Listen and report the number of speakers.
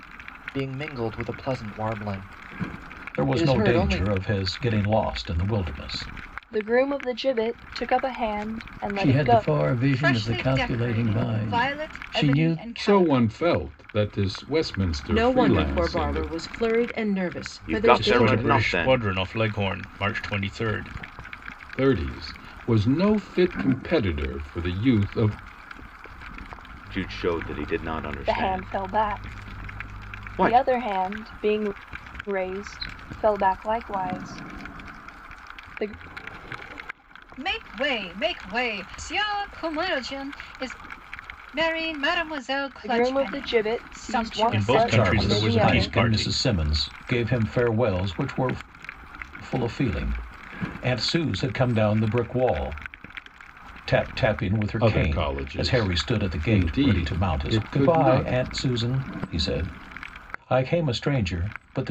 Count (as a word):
nine